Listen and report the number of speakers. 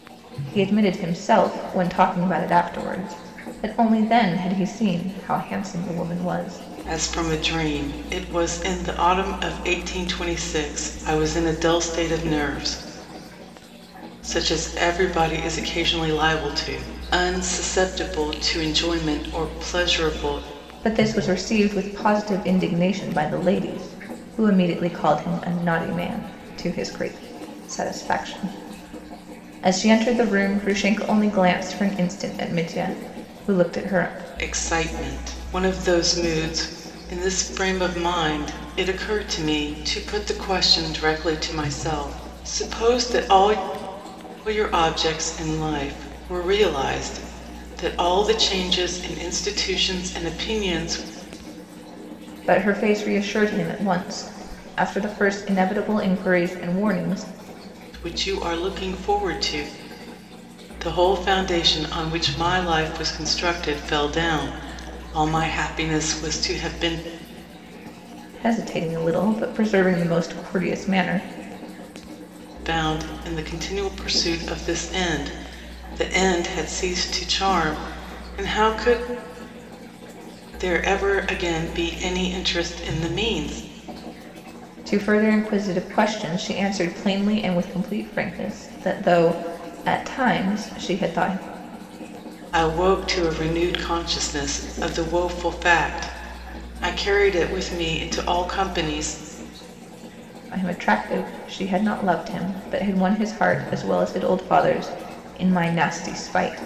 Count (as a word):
two